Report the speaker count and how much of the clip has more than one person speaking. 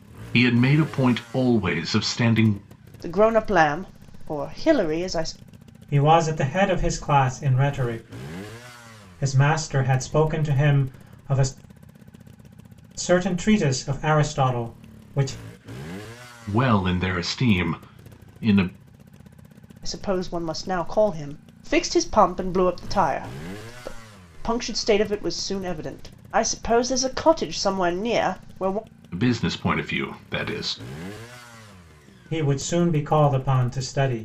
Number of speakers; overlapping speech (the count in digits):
3, no overlap